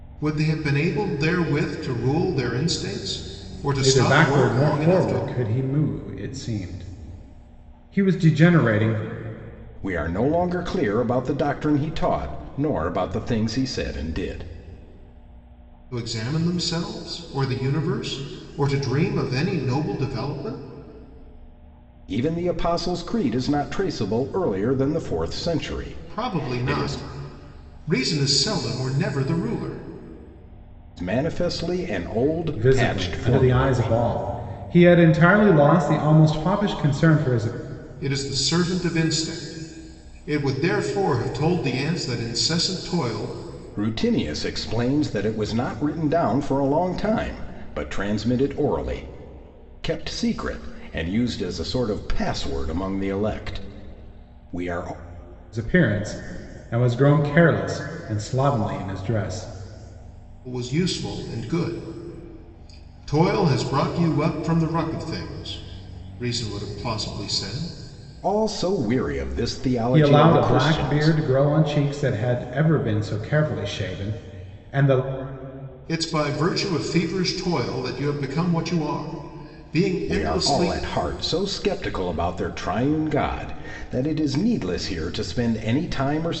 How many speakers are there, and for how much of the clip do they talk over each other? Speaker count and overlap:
3, about 7%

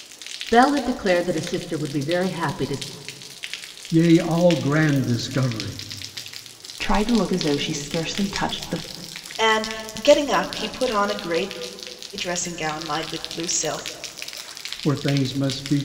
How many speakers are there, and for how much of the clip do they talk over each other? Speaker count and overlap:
4, no overlap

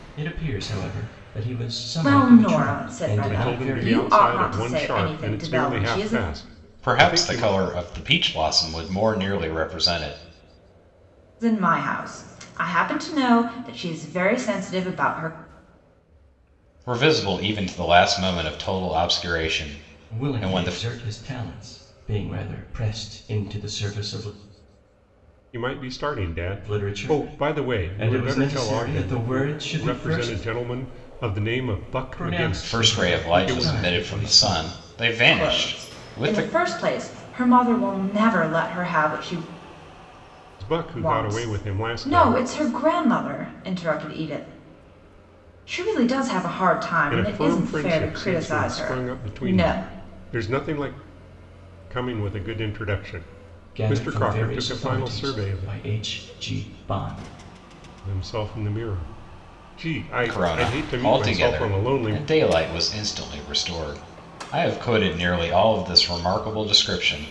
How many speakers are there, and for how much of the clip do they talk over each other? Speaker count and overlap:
4, about 32%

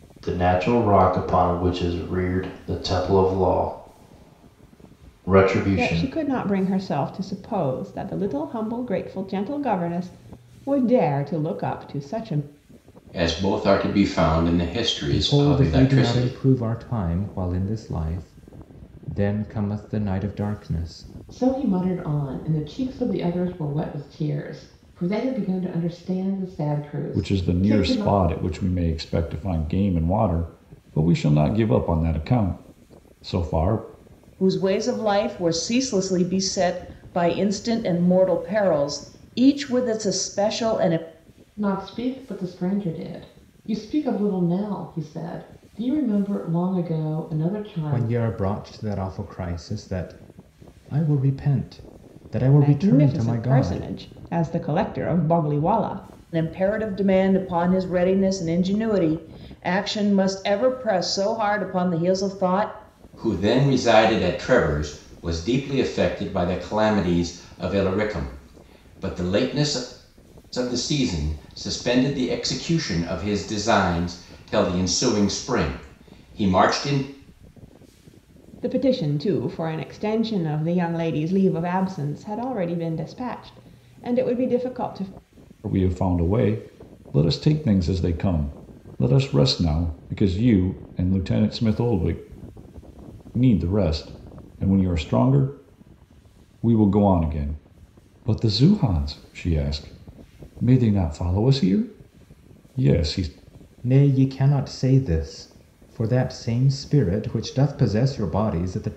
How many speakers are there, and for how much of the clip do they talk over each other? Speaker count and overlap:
7, about 4%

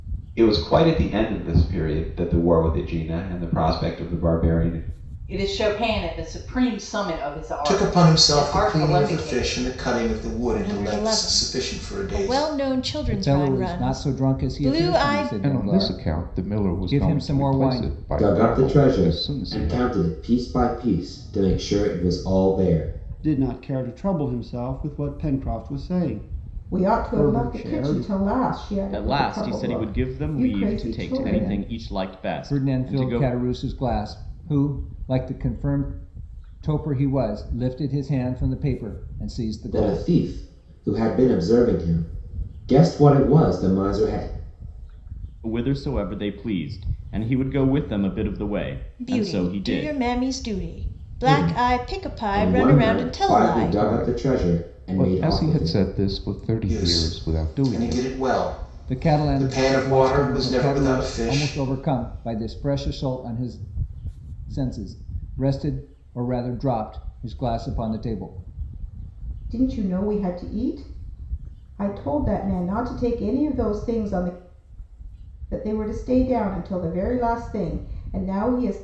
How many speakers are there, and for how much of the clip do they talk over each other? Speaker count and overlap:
10, about 34%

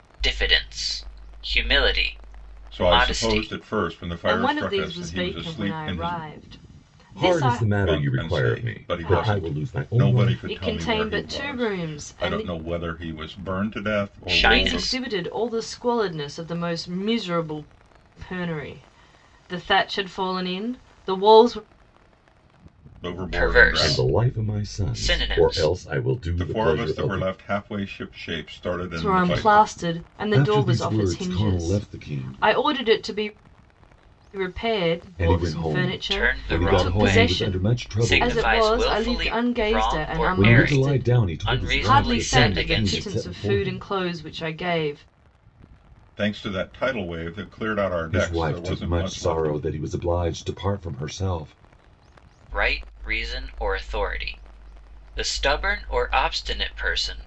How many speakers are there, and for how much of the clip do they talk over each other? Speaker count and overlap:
4, about 45%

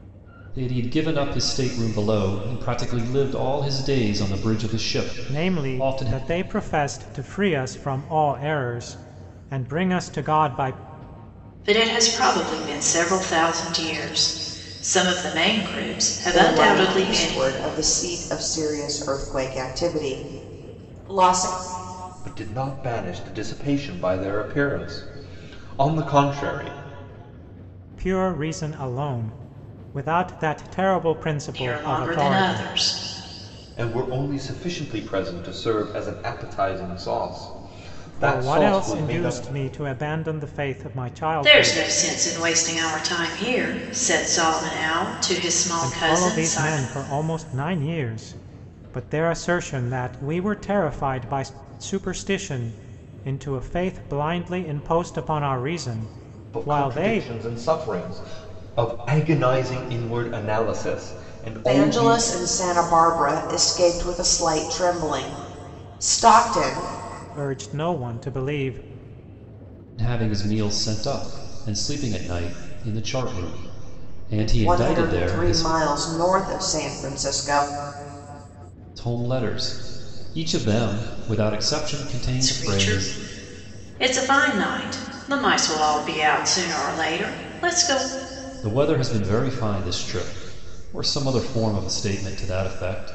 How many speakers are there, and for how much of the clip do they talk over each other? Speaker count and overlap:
5, about 10%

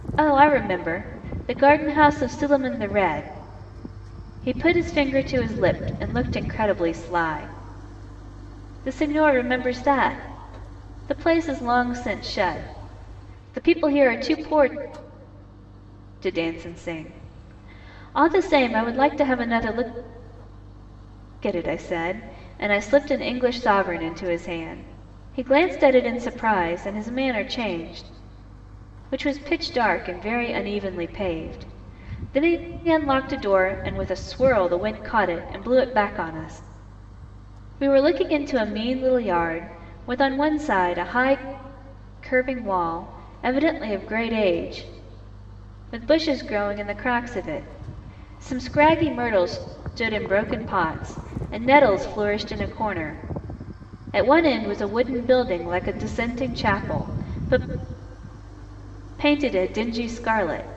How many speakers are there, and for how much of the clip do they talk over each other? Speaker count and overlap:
1, no overlap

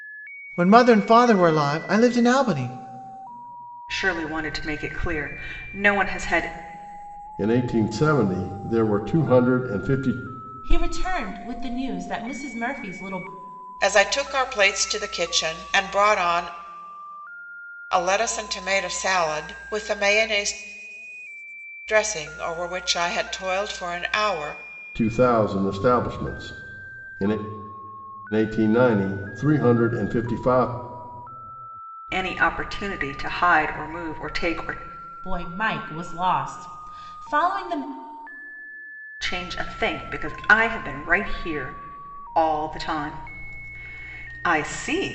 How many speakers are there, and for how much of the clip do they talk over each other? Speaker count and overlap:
5, no overlap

